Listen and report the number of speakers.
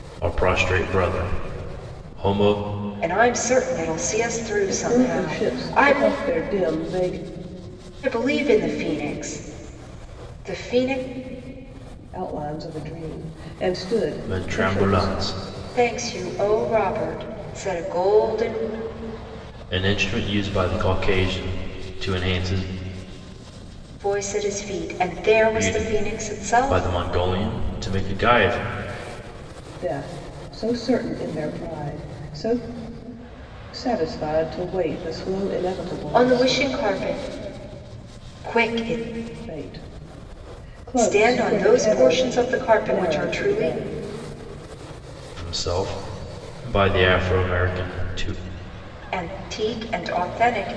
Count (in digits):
3